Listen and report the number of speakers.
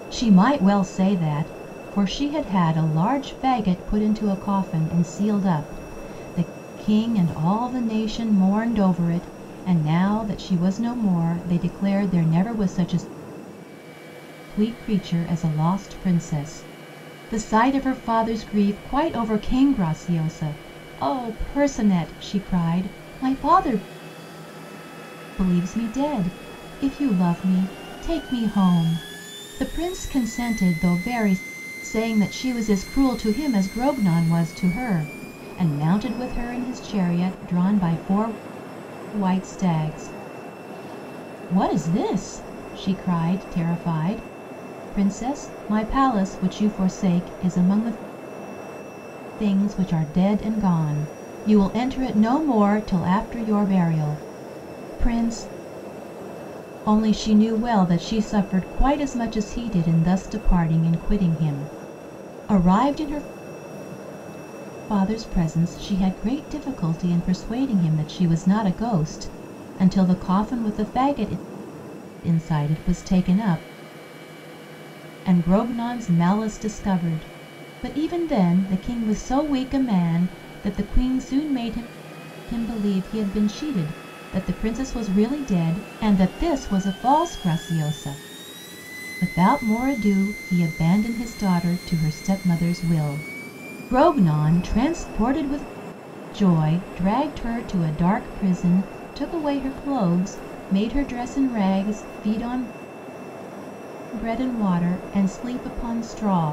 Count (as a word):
one